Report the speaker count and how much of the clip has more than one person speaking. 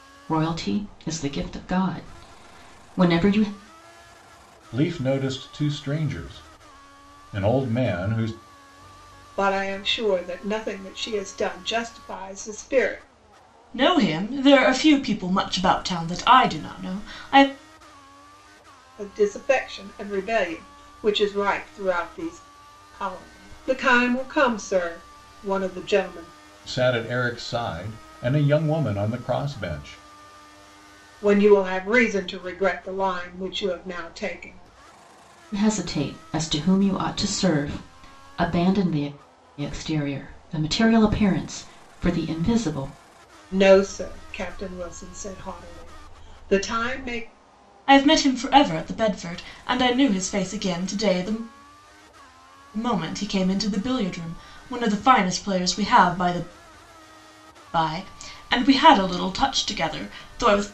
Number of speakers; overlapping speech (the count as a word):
four, no overlap